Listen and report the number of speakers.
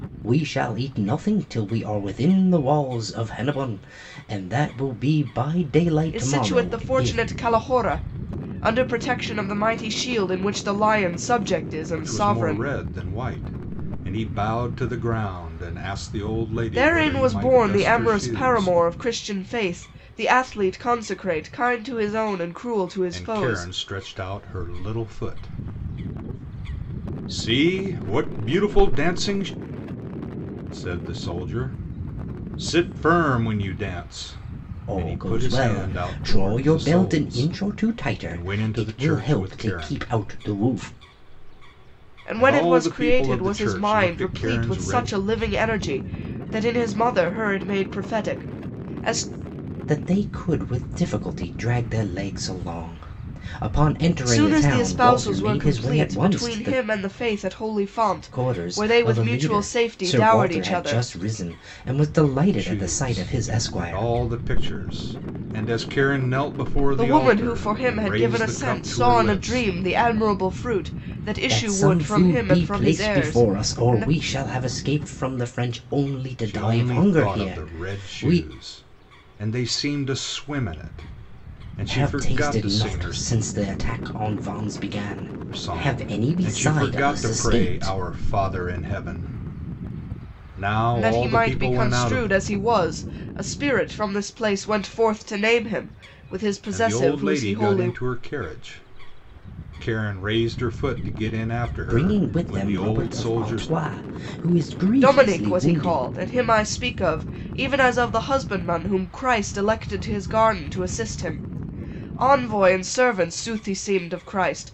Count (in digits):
3